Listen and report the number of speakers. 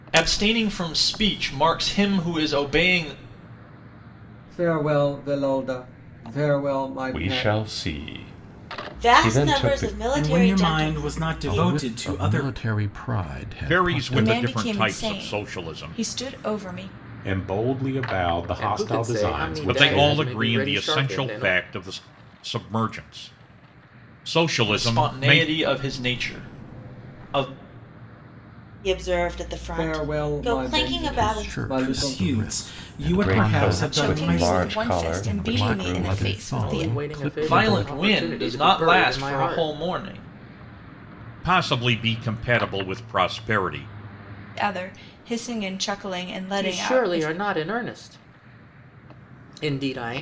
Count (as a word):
ten